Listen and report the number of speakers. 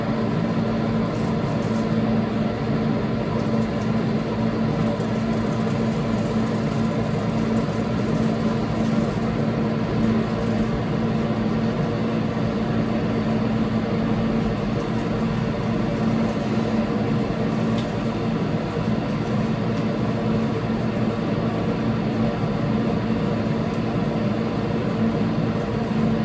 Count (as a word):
zero